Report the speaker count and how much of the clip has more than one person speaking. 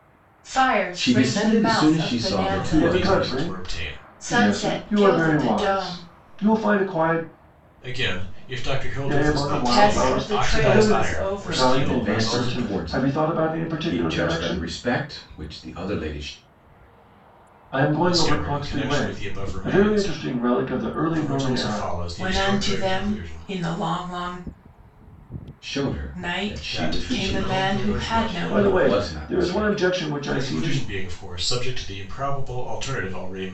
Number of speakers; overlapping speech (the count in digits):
4, about 56%